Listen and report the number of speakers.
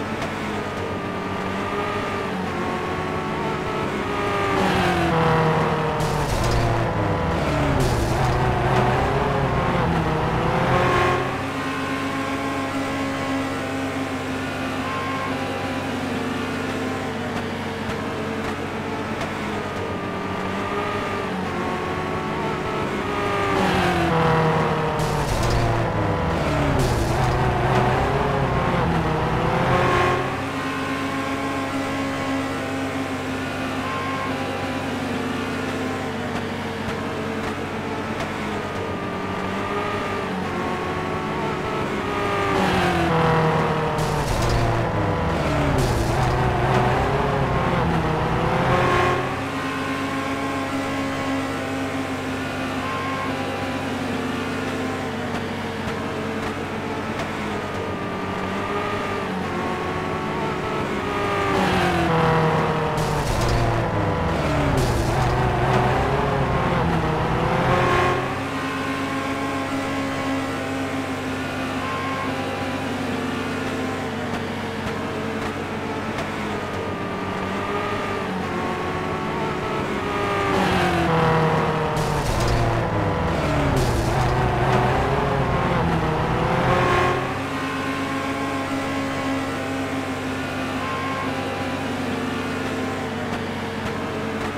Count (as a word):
zero